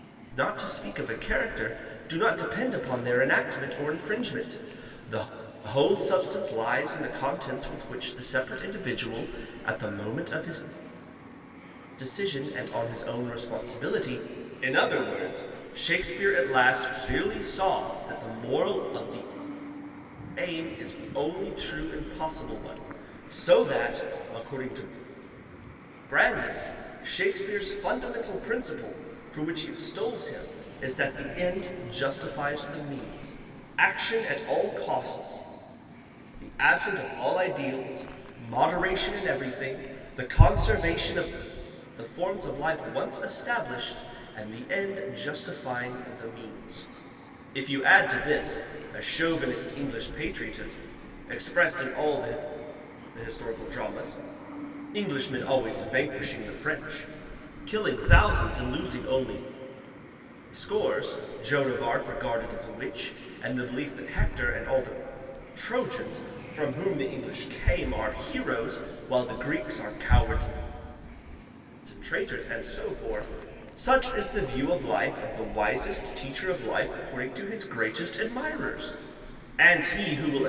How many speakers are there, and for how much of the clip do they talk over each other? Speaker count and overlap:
one, no overlap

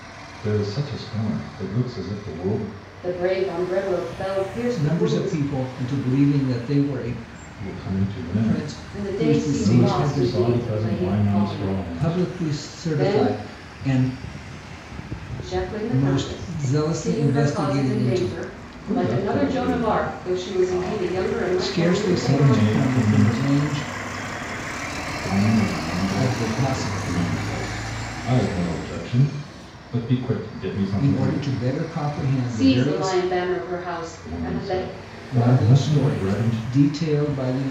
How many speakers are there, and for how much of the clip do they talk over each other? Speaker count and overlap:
three, about 47%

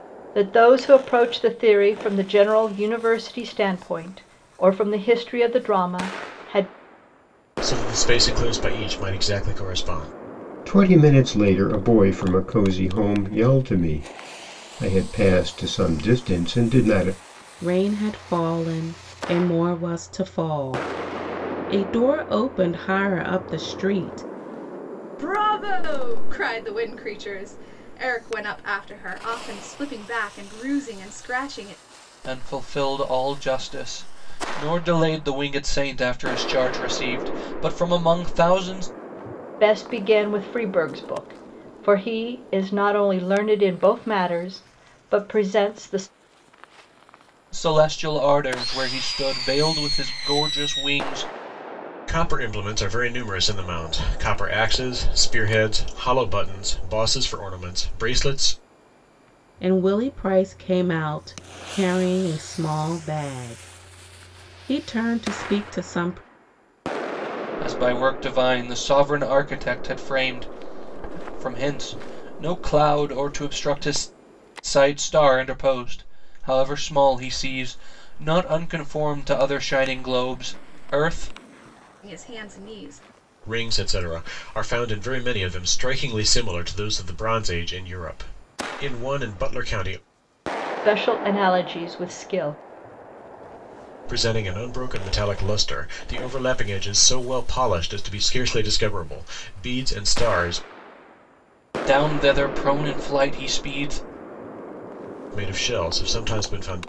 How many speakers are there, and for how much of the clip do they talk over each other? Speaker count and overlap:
six, no overlap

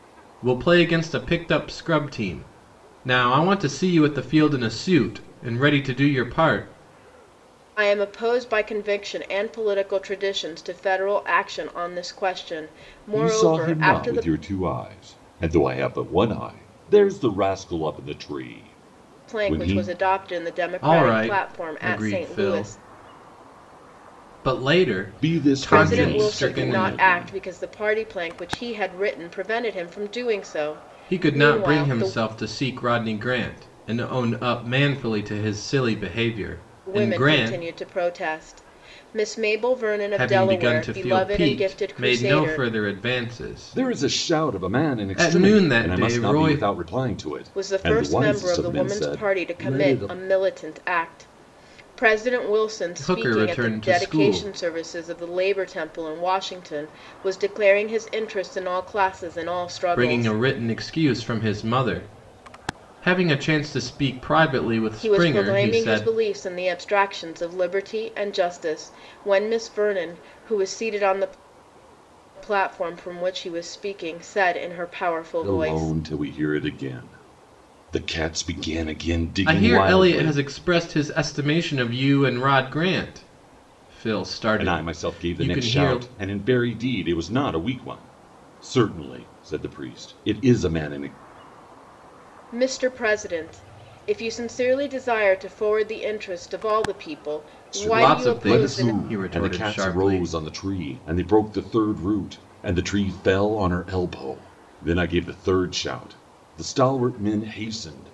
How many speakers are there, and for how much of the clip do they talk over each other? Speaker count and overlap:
three, about 23%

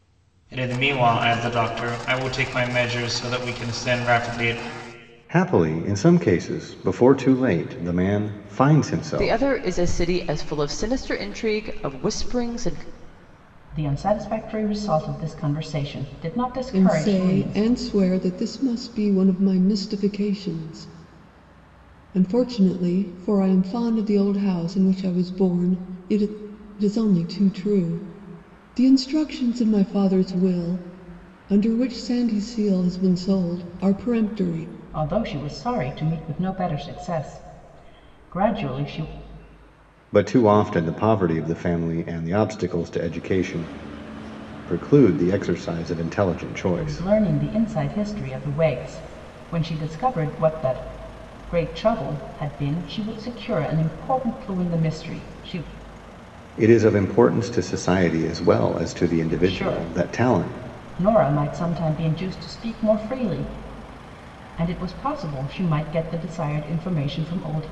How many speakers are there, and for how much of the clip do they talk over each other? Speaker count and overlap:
five, about 4%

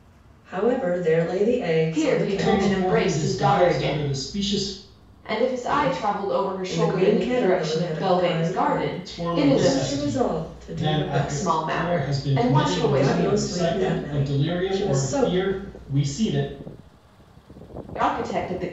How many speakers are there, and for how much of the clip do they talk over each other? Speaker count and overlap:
three, about 63%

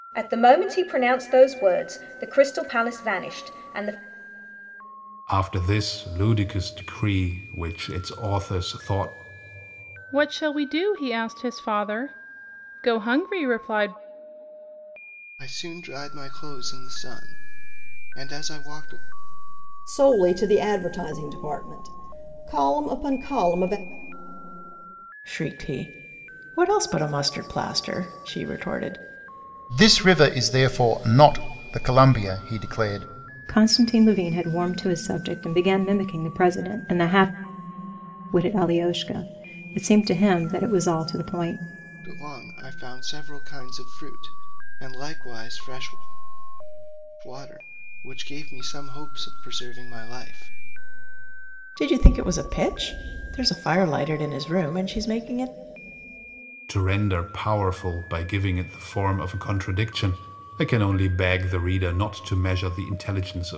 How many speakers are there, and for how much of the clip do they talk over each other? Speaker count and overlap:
eight, no overlap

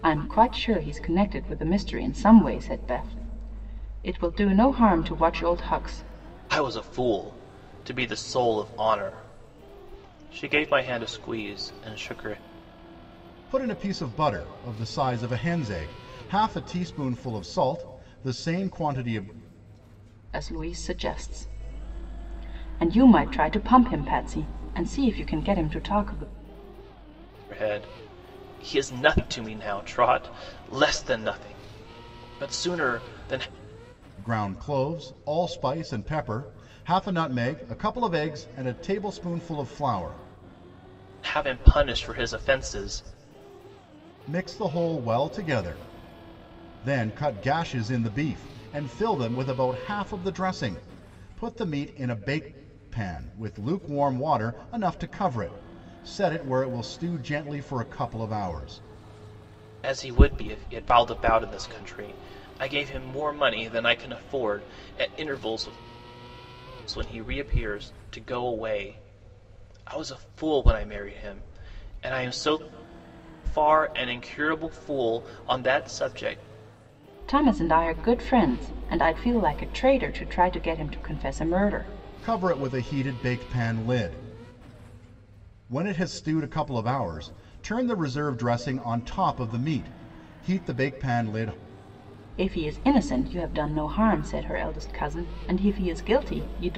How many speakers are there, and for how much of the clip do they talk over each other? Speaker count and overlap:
three, no overlap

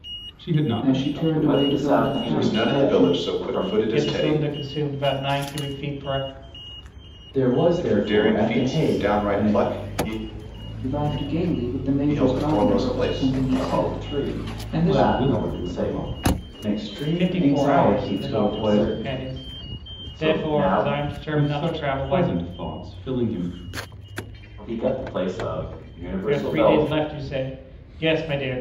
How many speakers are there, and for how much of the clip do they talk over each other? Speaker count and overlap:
six, about 49%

